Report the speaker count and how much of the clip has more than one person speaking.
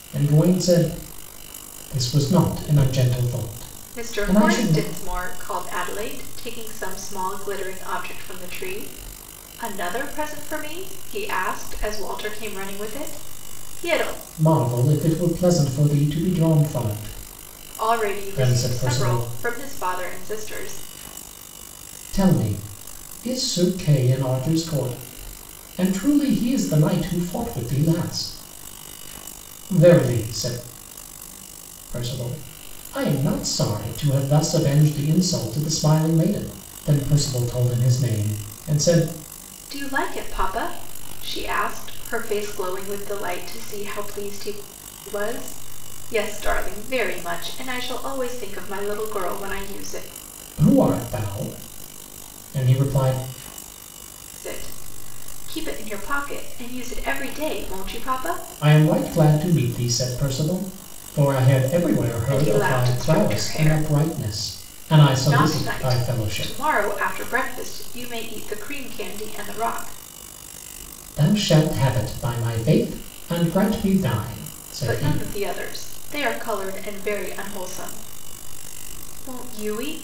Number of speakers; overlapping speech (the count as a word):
two, about 7%